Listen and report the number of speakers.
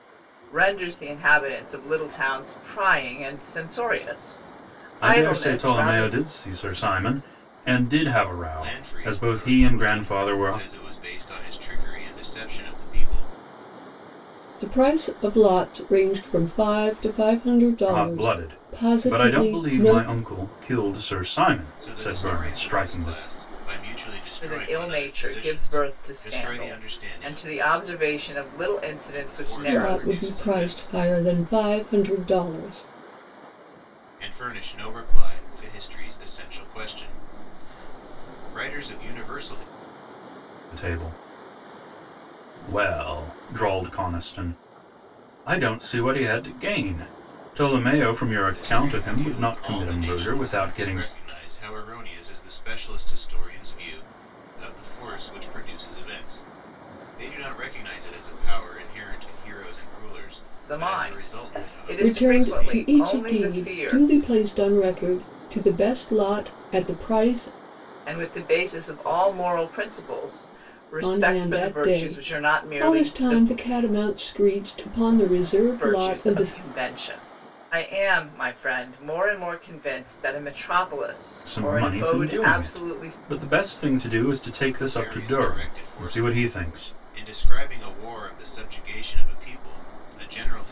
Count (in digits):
4